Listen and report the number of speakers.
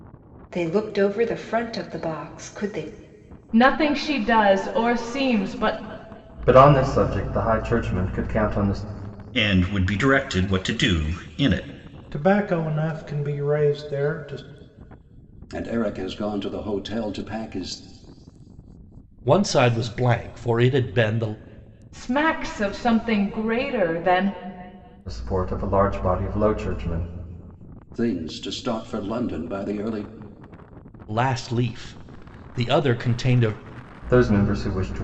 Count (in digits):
7